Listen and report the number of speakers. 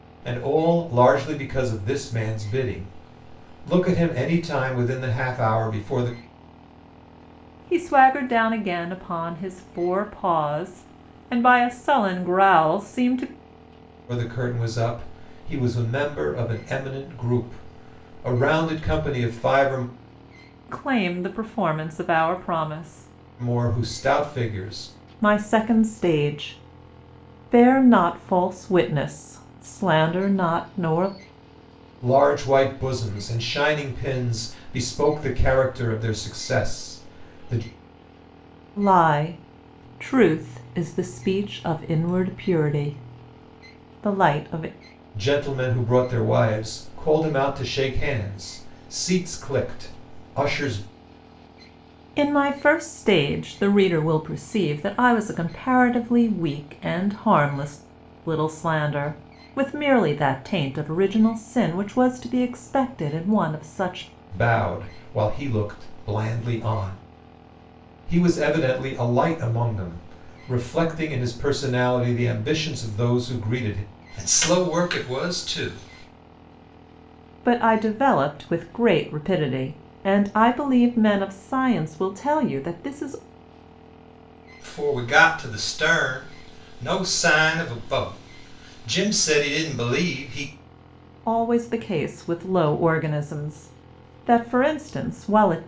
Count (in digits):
2